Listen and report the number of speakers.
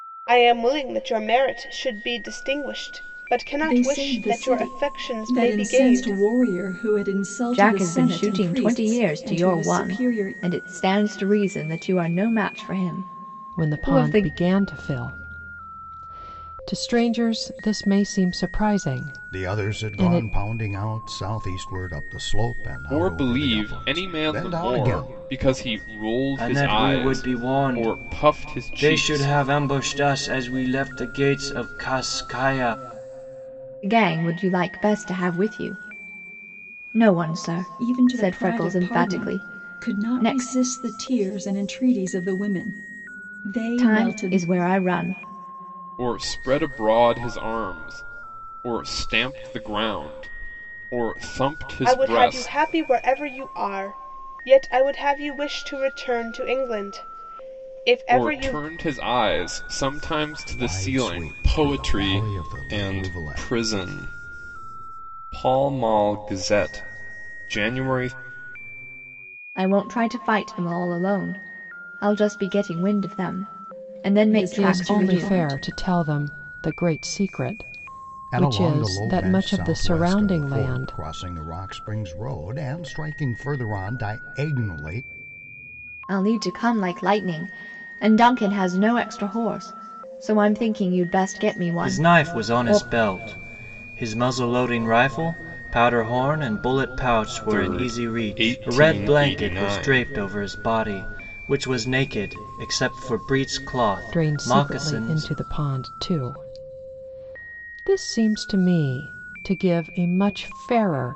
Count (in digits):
7